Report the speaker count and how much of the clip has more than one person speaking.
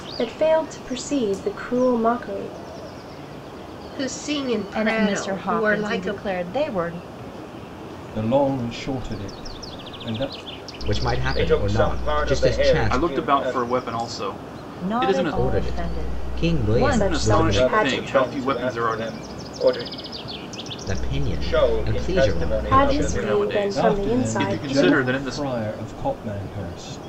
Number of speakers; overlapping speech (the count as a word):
seven, about 45%